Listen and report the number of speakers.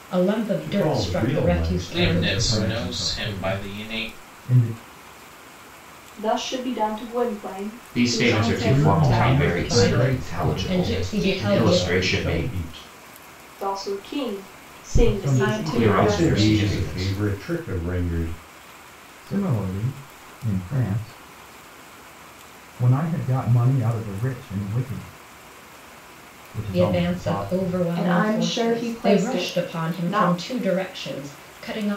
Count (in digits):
7